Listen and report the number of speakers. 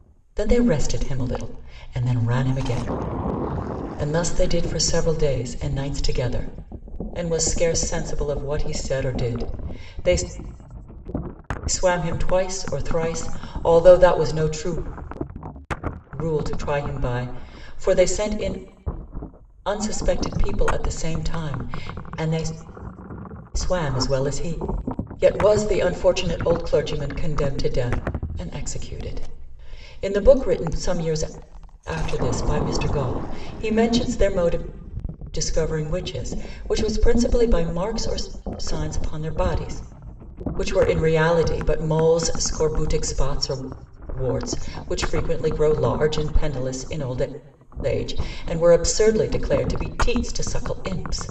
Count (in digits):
1